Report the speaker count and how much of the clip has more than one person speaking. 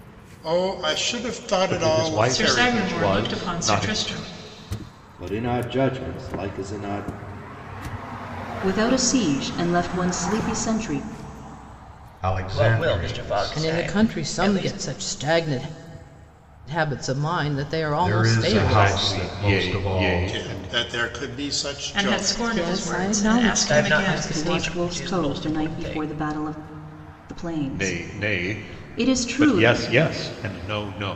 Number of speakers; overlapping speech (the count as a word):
eight, about 44%